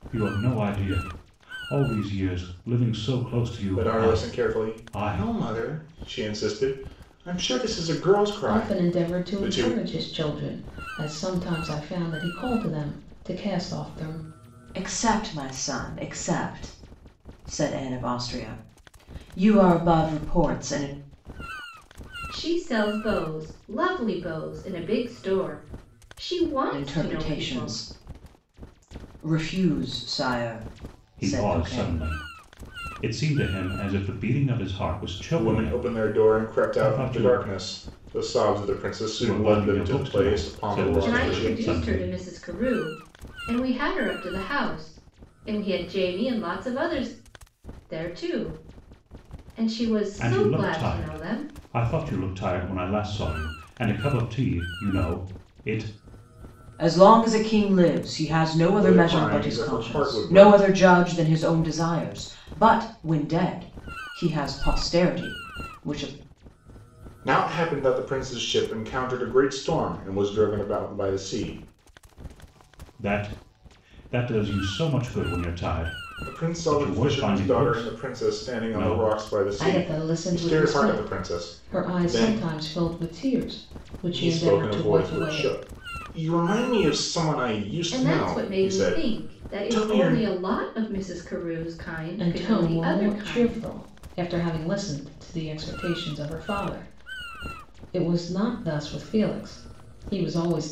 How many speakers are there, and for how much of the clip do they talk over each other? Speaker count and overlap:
five, about 23%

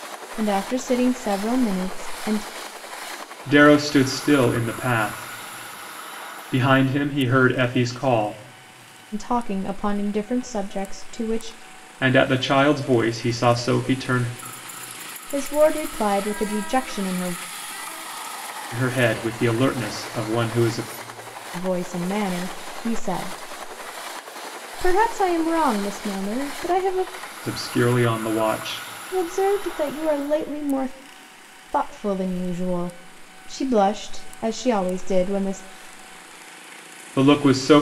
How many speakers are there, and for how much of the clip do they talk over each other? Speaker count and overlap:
two, no overlap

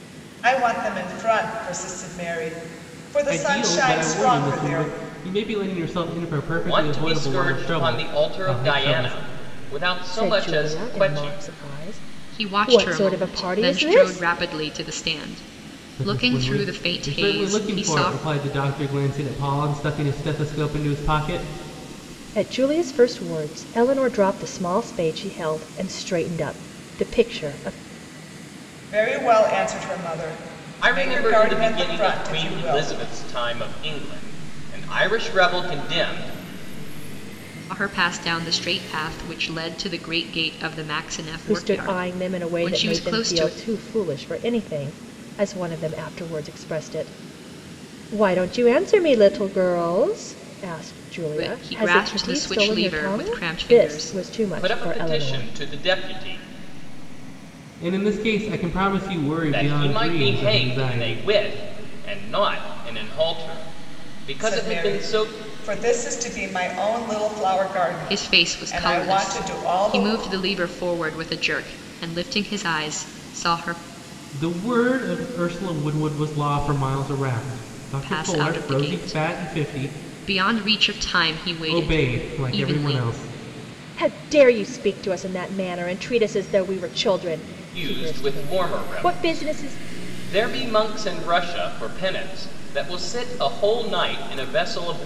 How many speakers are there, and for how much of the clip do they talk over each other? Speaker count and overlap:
five, about 29%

